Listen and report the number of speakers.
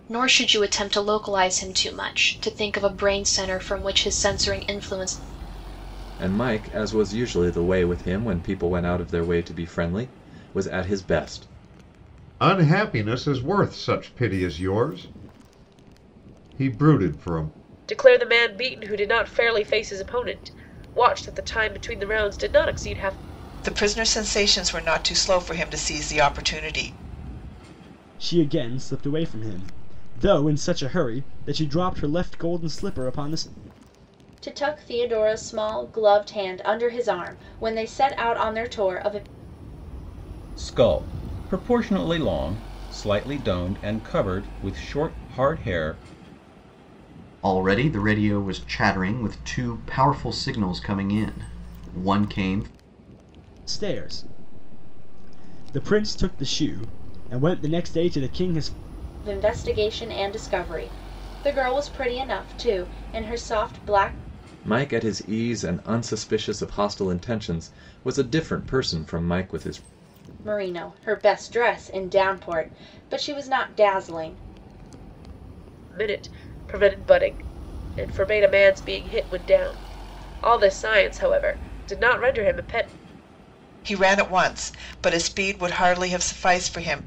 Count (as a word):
nine